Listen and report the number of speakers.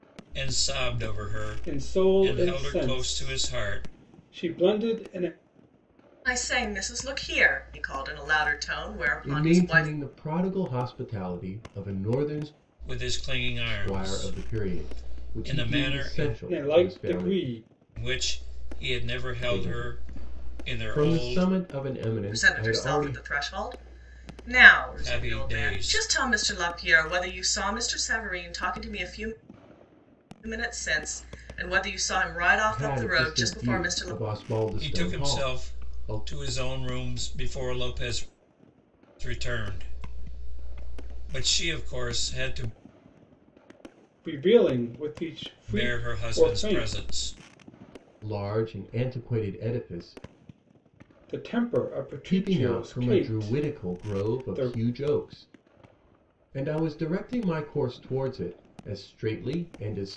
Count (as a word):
four